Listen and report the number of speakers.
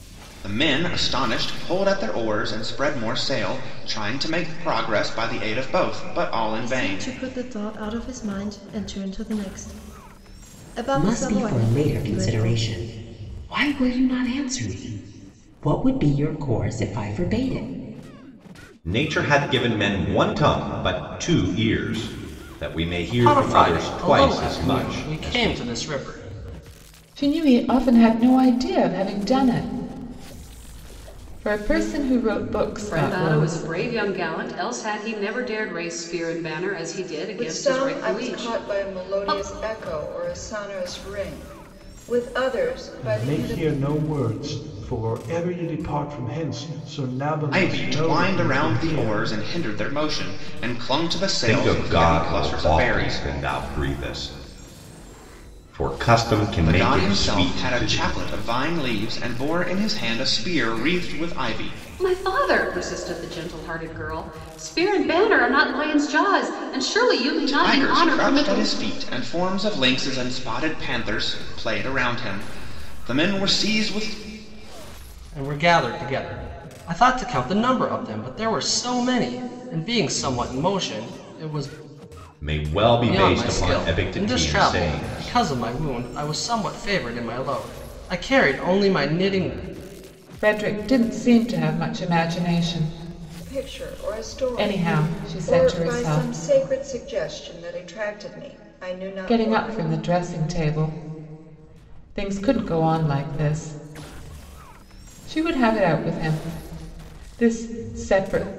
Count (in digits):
9